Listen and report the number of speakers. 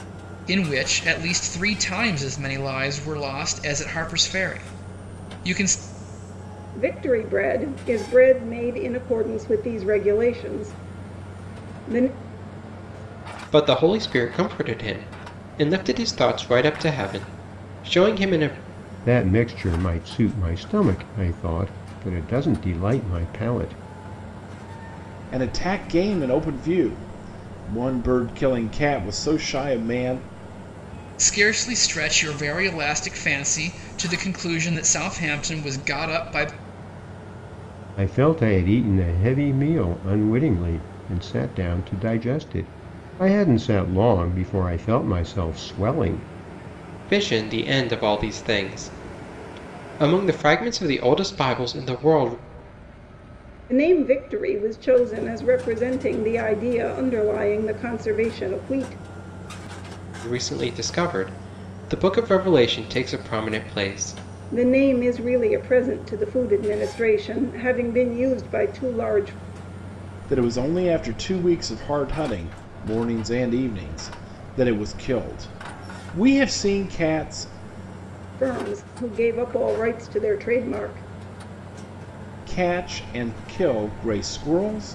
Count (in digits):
5